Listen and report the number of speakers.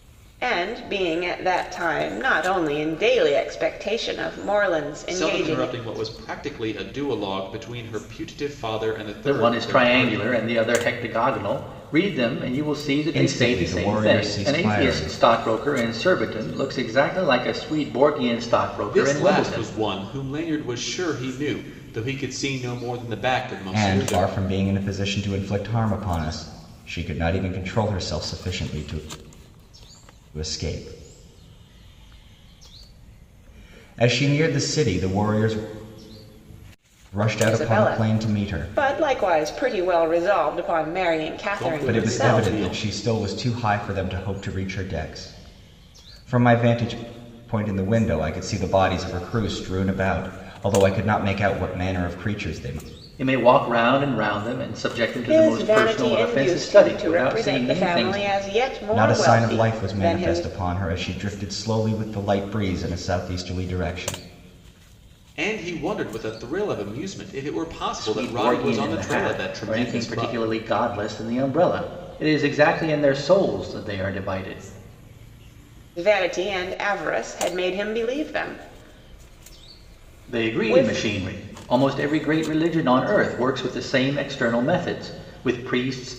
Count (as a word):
four